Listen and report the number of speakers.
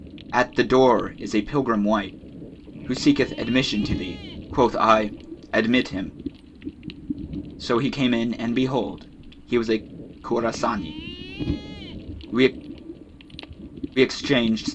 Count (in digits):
1